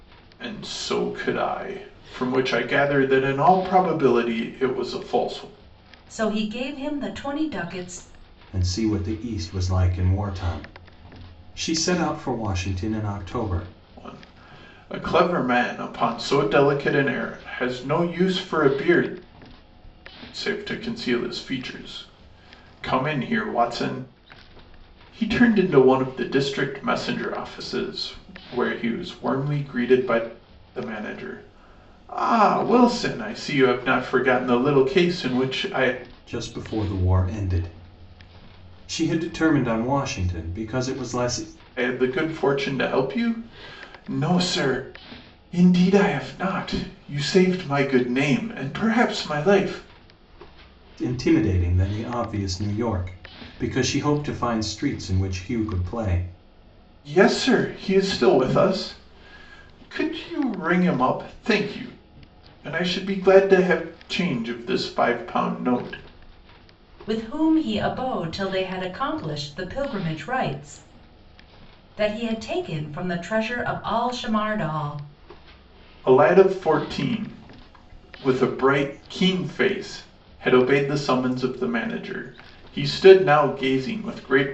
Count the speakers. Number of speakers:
three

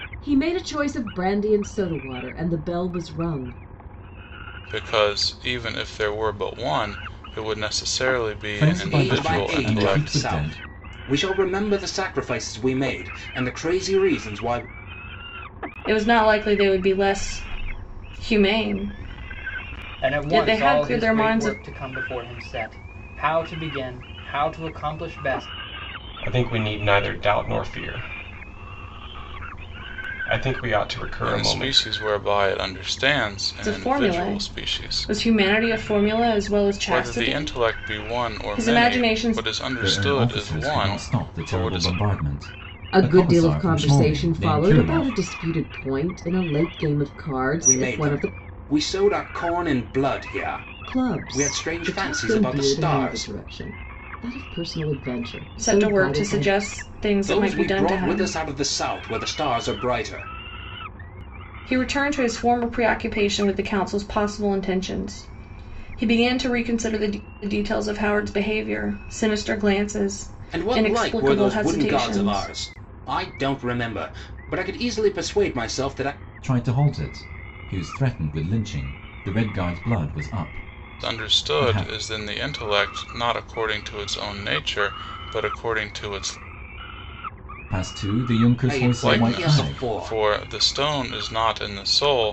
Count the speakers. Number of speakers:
seven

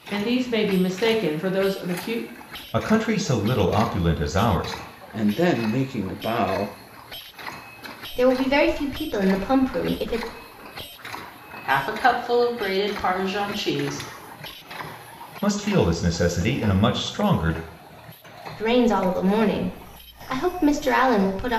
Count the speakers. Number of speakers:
five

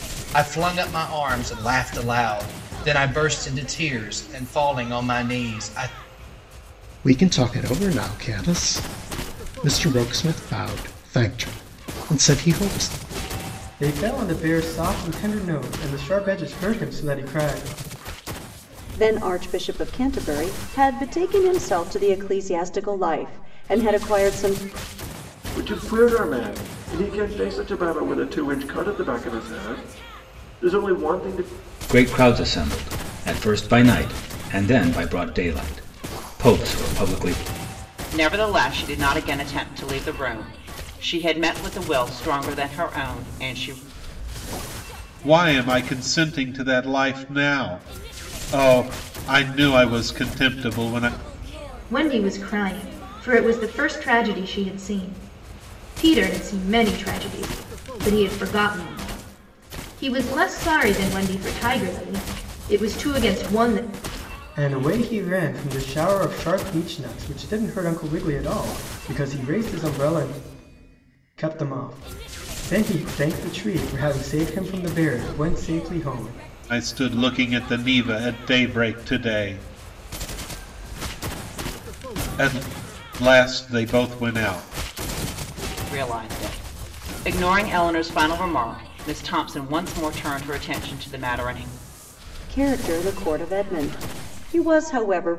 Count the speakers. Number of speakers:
nine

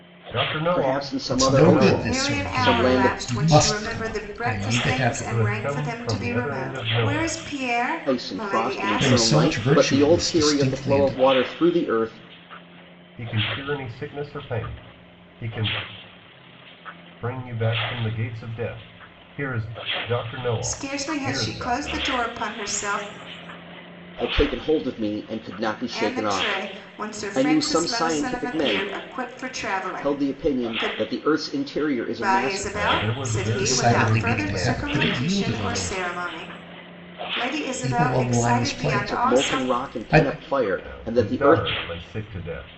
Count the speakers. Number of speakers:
four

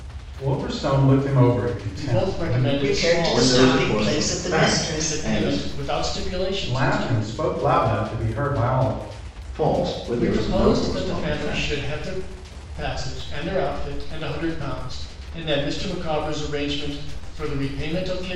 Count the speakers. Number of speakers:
four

